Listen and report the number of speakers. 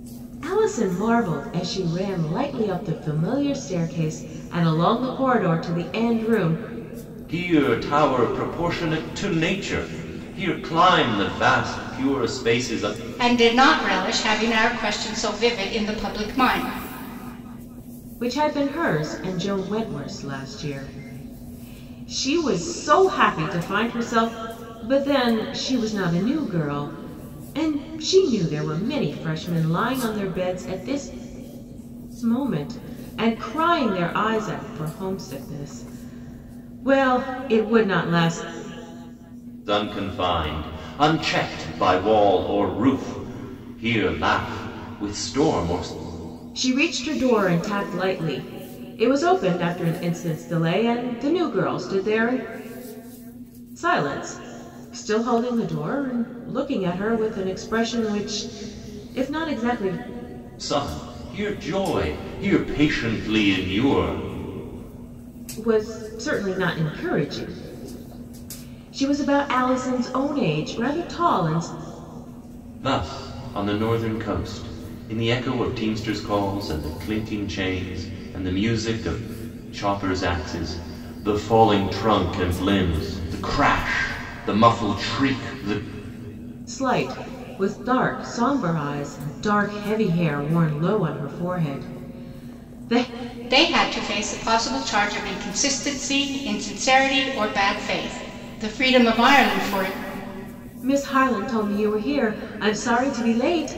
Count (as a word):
three